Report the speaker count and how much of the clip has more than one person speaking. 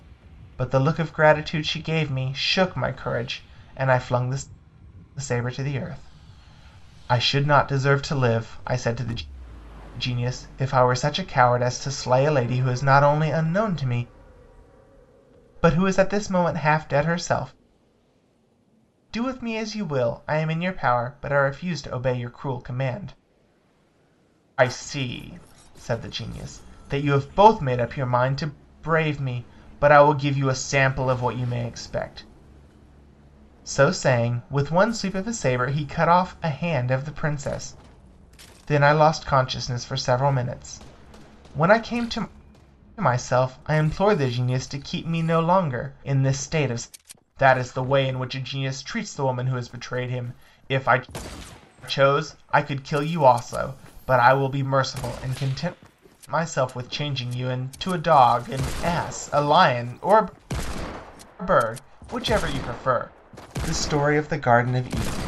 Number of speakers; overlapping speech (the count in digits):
1, no overlap